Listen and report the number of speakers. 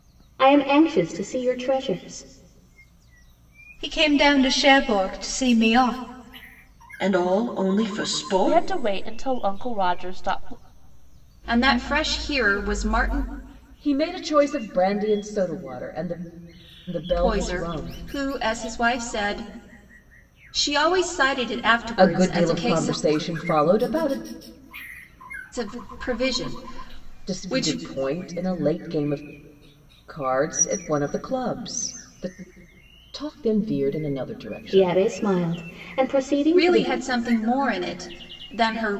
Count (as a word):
six